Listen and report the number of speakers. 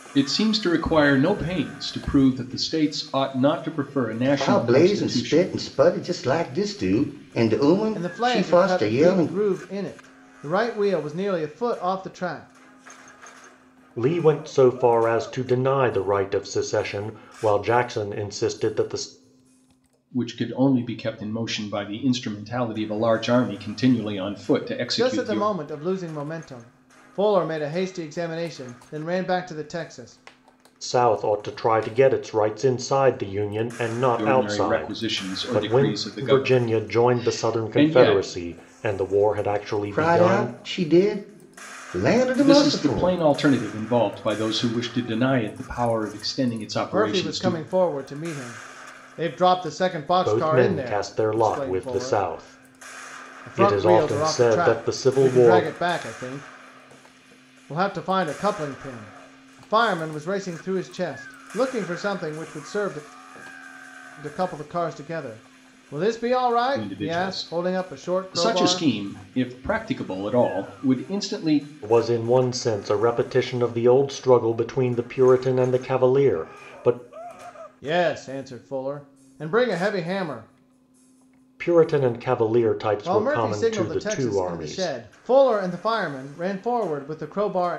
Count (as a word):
four